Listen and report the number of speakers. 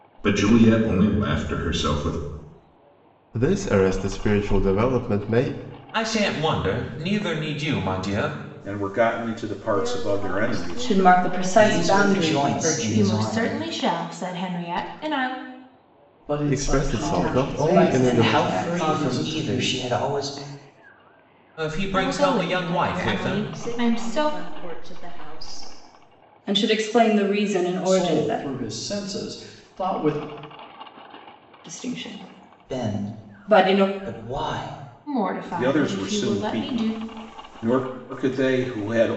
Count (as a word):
nine